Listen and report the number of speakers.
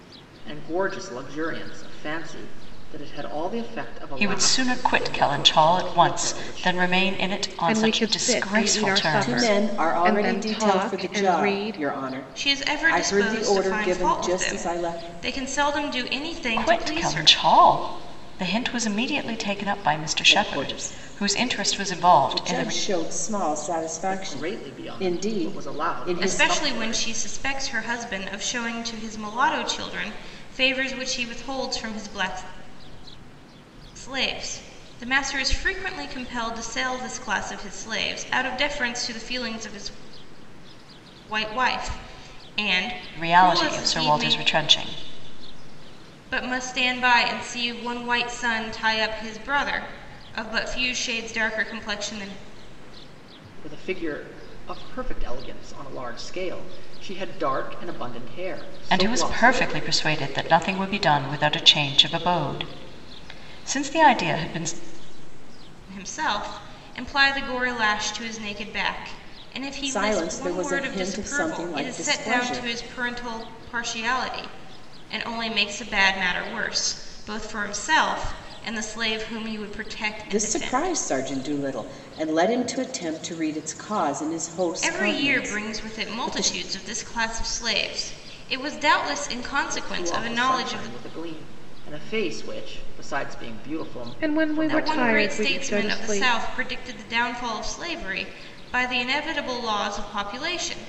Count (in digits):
5